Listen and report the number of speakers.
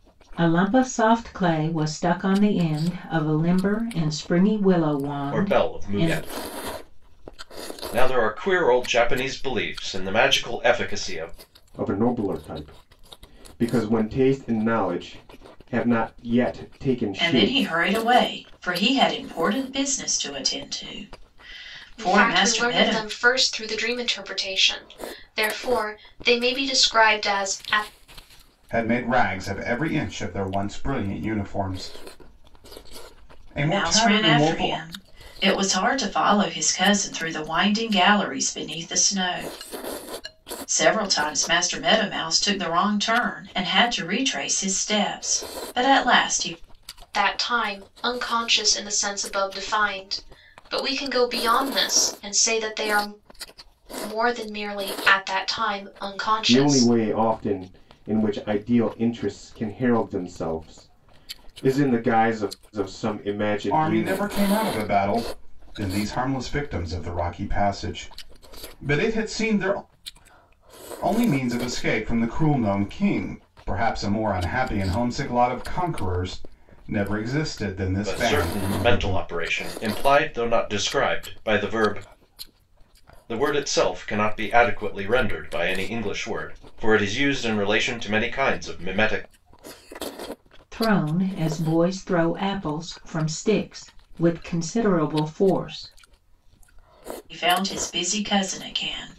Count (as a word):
six